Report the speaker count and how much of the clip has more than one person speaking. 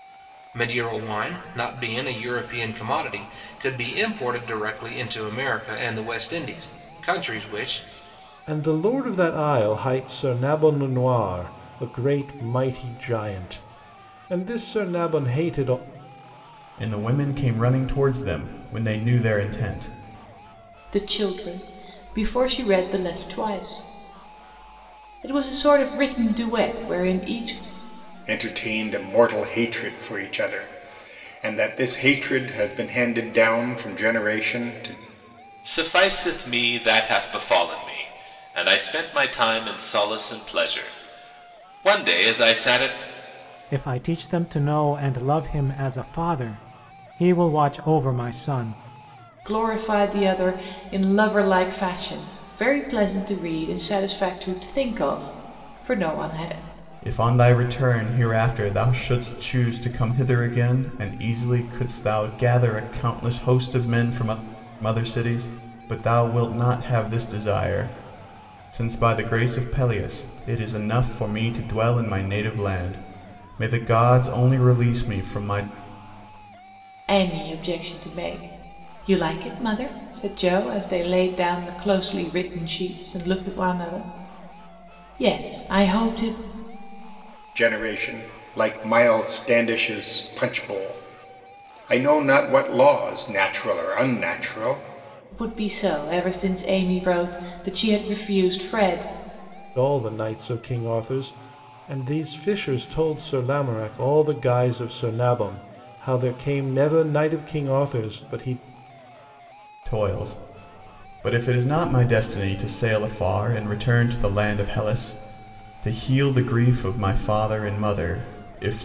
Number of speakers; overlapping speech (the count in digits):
7, no overlap